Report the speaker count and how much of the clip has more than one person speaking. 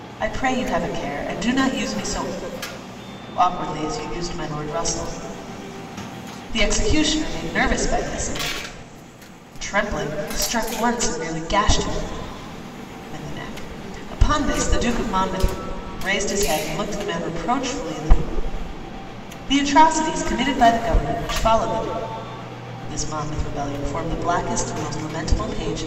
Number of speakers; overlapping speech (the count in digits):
1, no overlap